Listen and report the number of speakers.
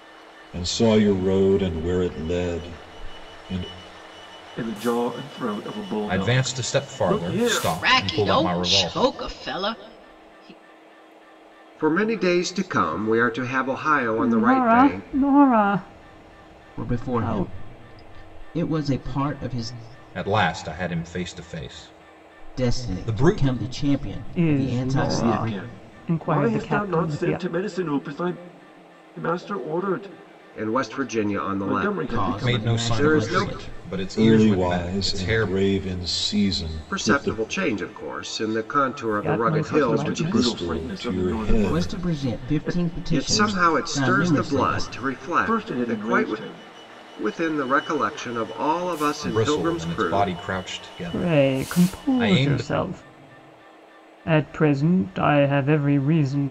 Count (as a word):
seven